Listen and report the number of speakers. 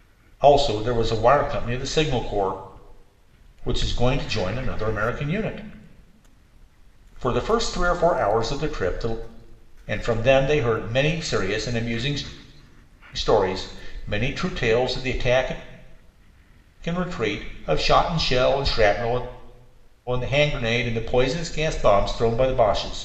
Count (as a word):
one